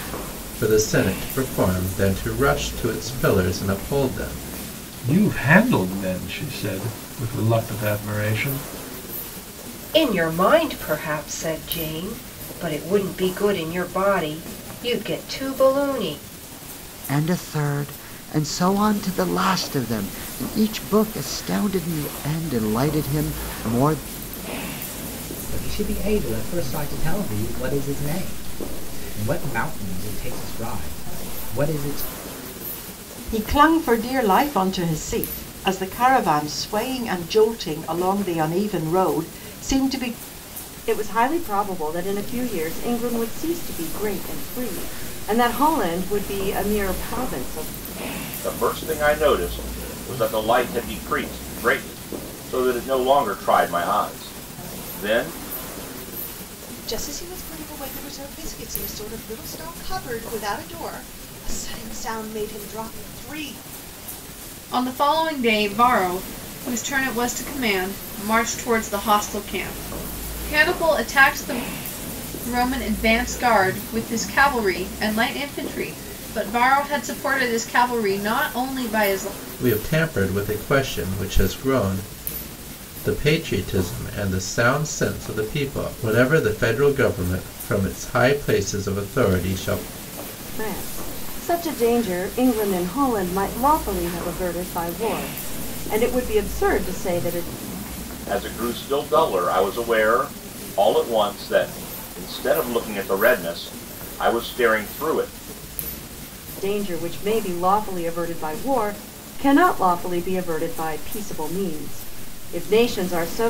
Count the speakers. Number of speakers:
10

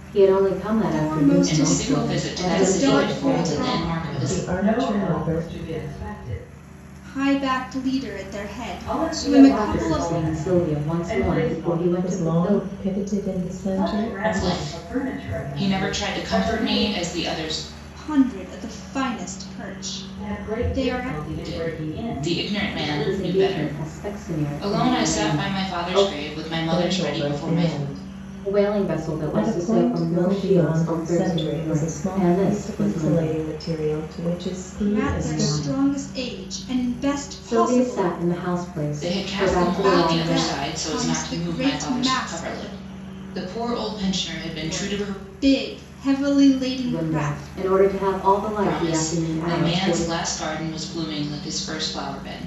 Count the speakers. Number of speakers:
5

